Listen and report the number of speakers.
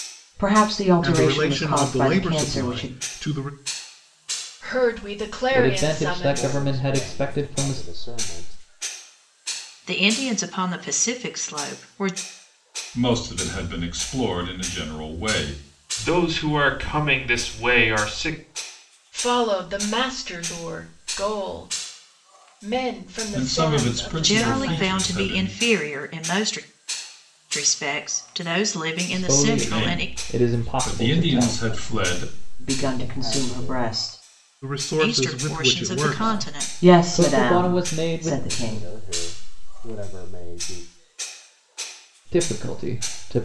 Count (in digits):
8